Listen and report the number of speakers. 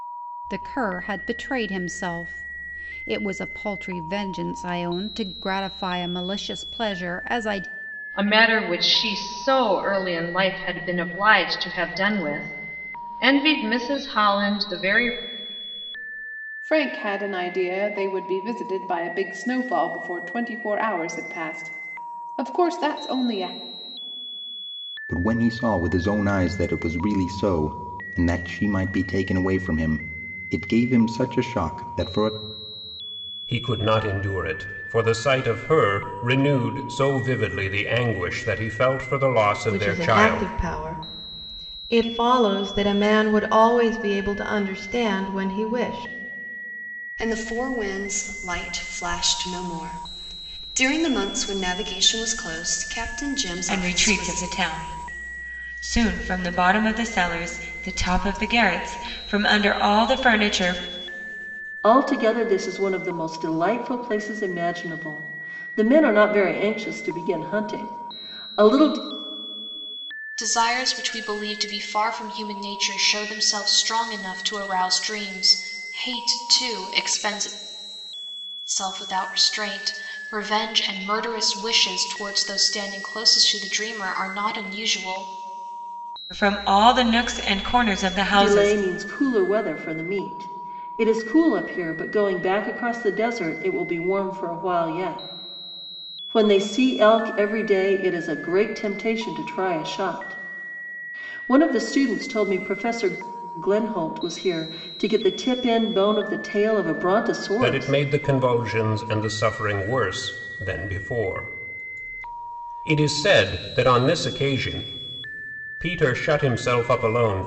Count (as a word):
ten